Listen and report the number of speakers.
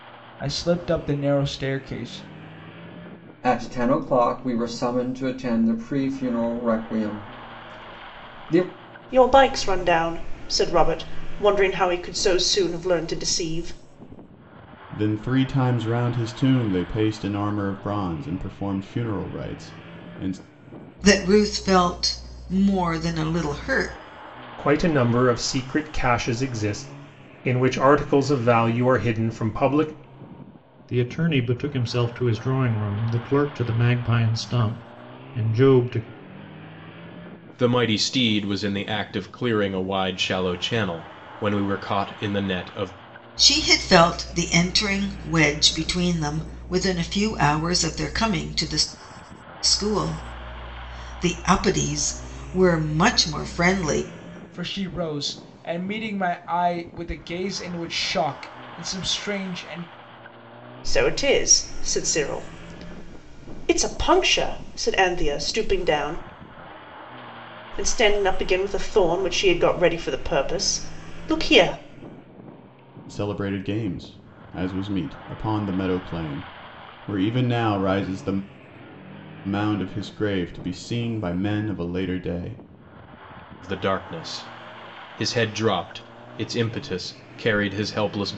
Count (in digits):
8